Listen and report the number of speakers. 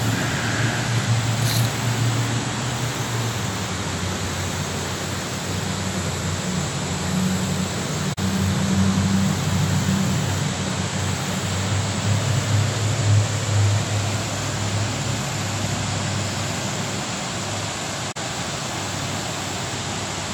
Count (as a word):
zero